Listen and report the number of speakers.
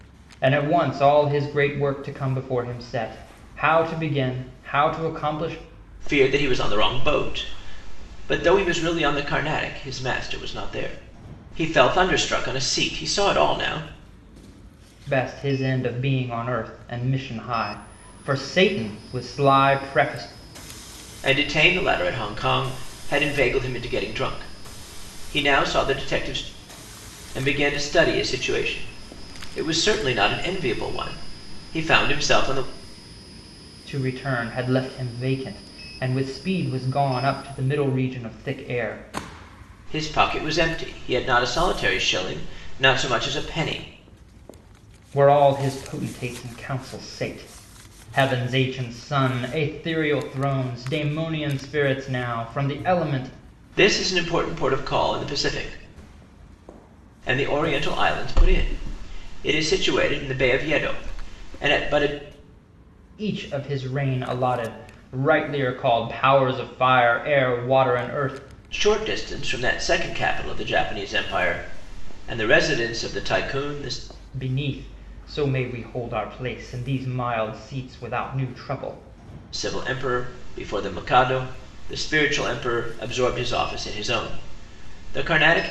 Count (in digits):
2